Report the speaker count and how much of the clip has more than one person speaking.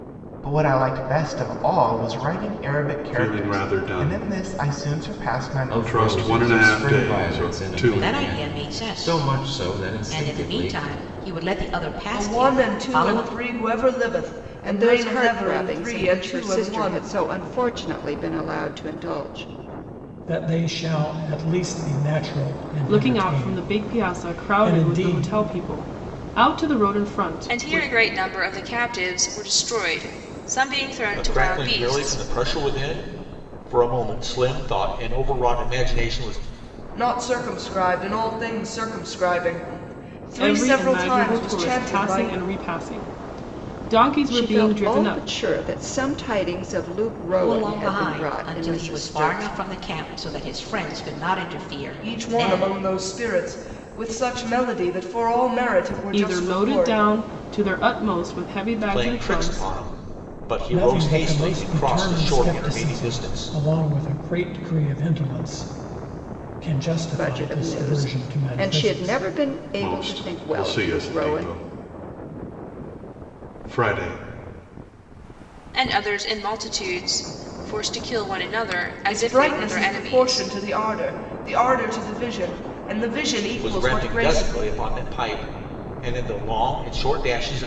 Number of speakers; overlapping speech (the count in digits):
10, about 37%